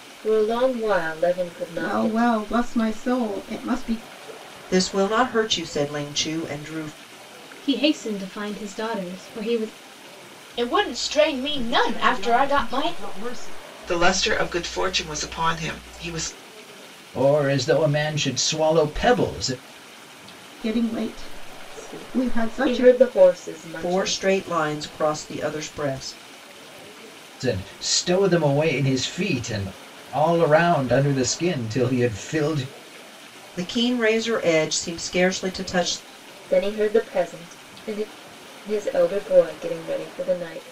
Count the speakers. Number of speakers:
8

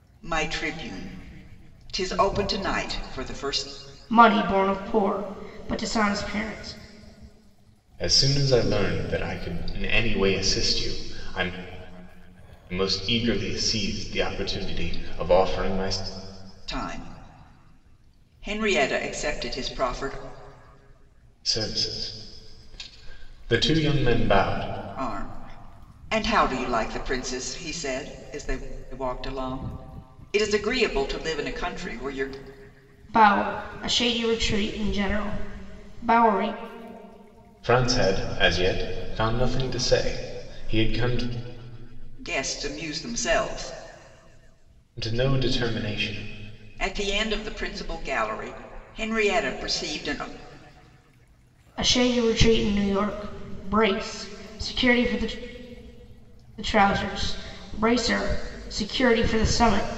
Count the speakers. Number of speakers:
3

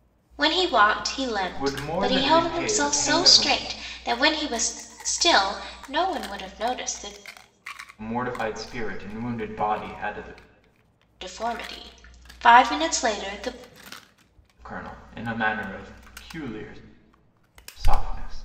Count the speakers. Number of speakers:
2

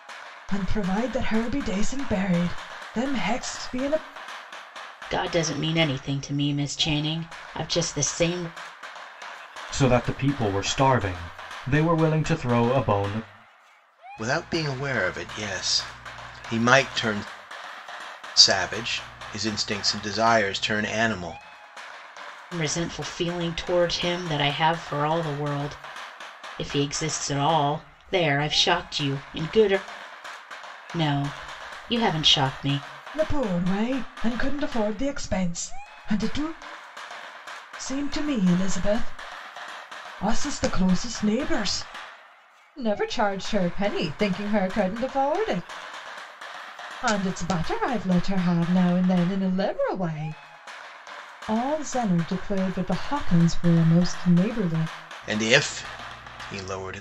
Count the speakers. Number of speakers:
4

